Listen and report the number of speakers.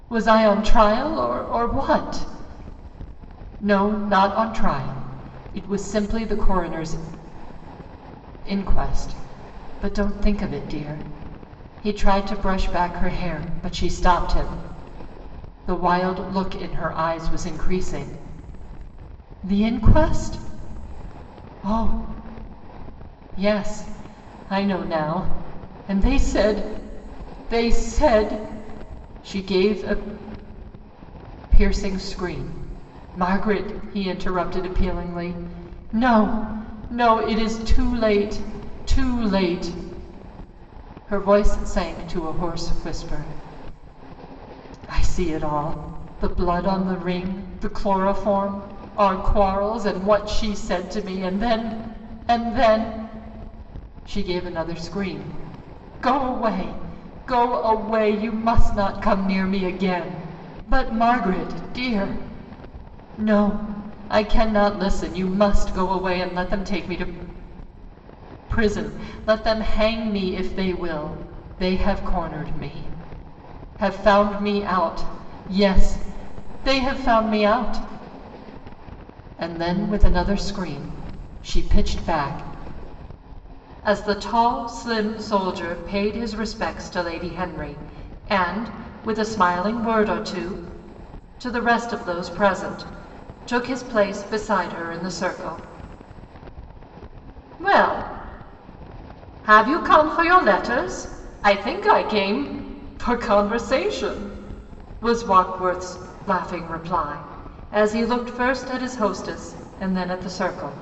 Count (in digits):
1